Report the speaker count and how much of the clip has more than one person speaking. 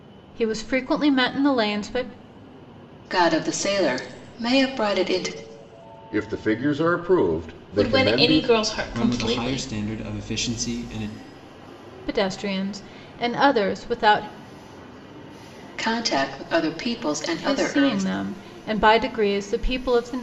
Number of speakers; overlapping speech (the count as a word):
five, about 11%